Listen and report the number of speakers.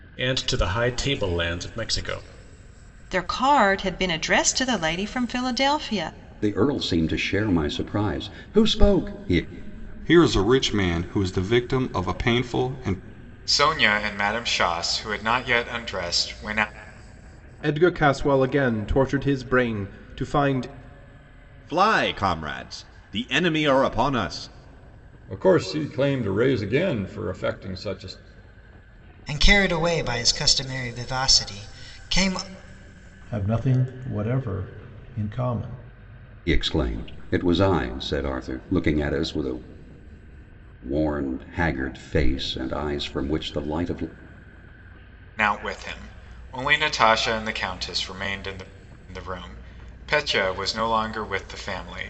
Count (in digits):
10